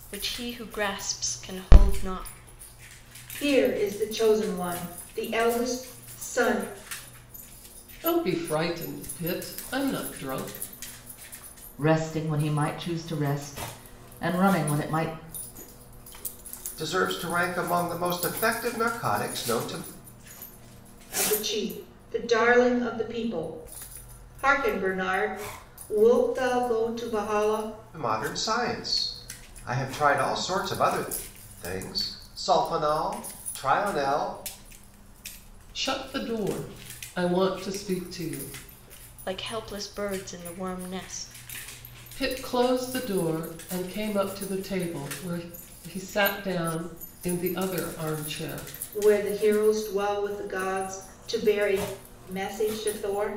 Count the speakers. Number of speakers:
five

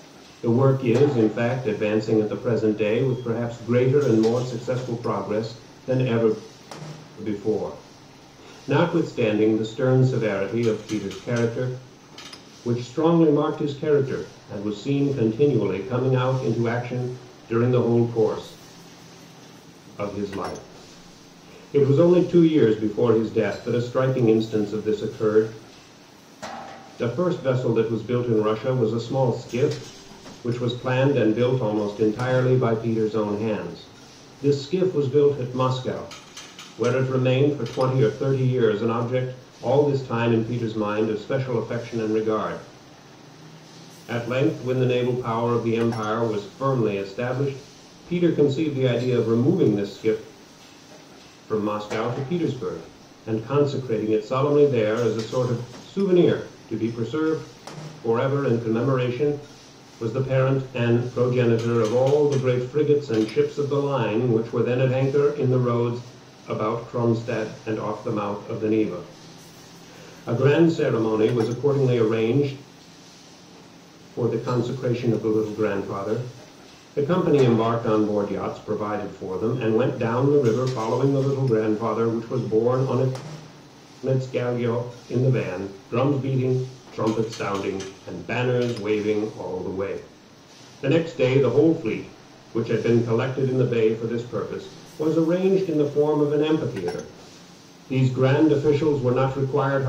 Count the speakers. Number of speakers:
one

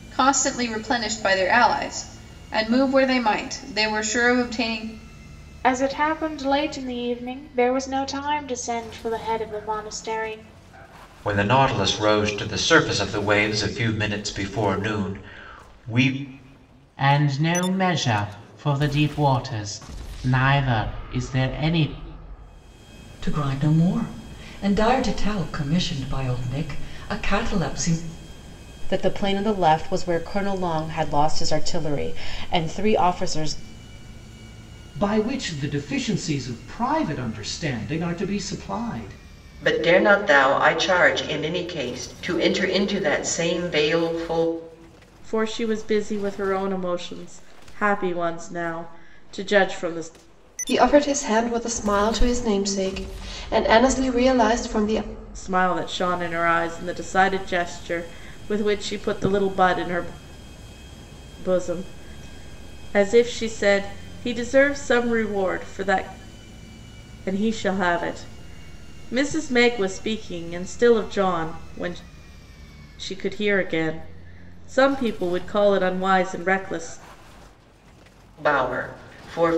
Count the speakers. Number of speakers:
ten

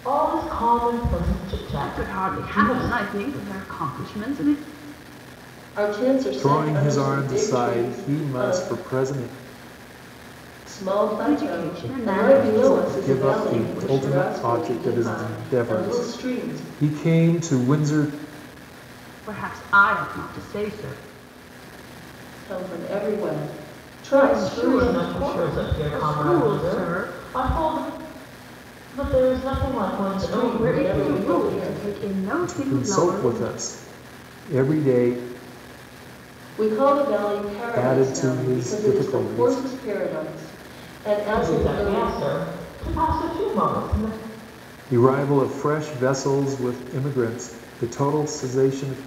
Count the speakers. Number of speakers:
four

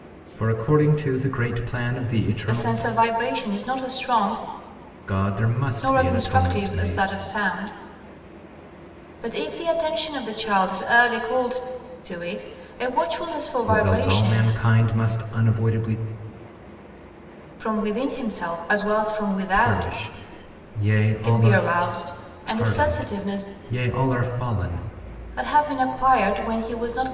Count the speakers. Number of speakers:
two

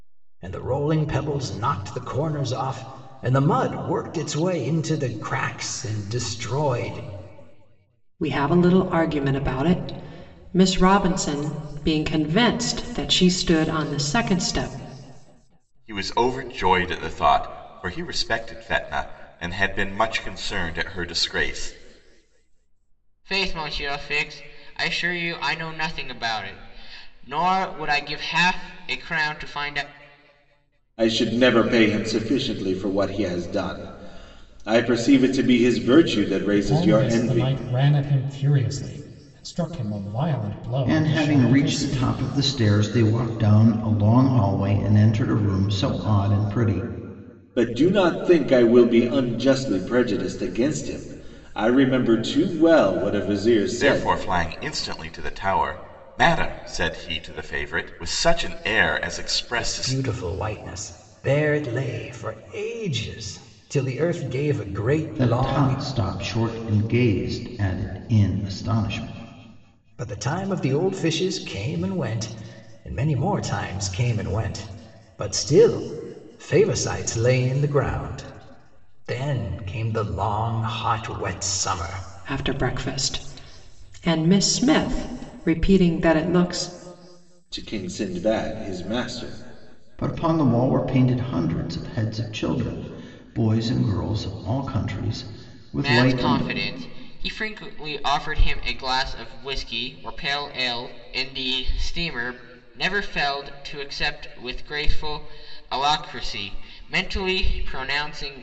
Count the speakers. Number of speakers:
seven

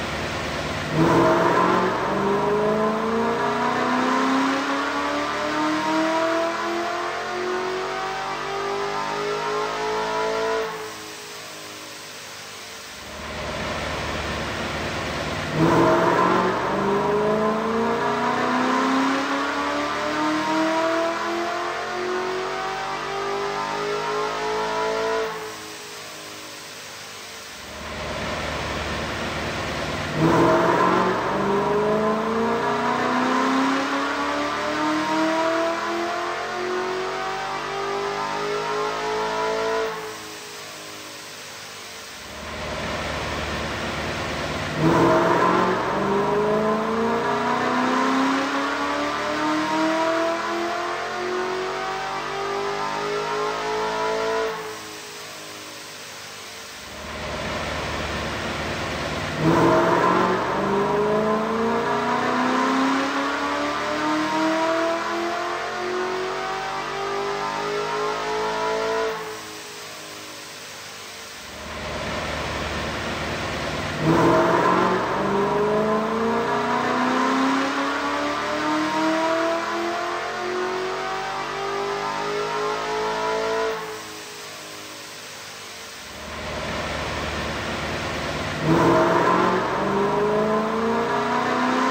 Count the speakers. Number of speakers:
zero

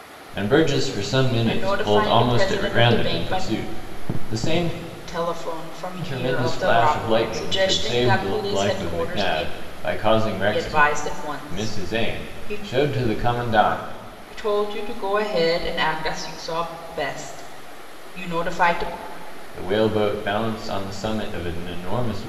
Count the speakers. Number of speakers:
two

